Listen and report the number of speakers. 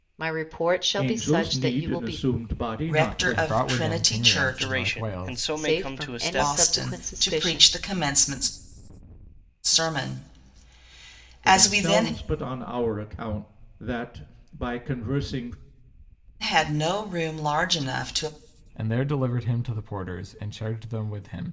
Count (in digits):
5